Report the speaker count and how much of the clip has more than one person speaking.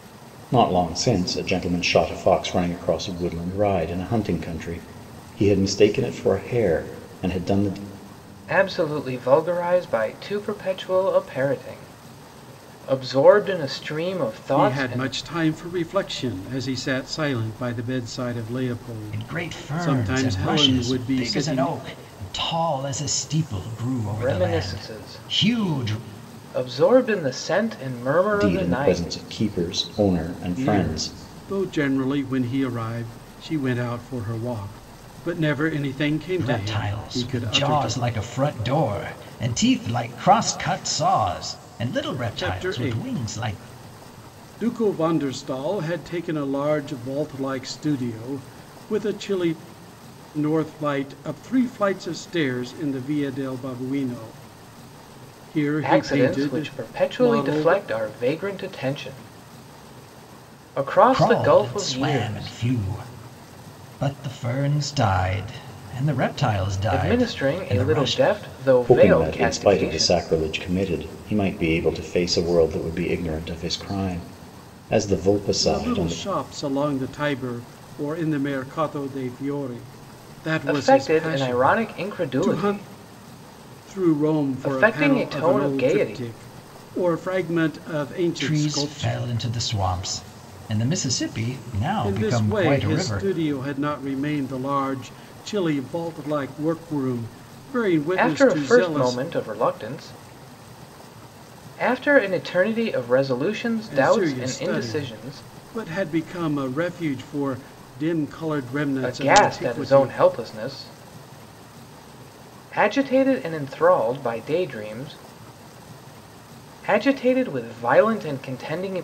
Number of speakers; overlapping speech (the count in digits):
4, about 23%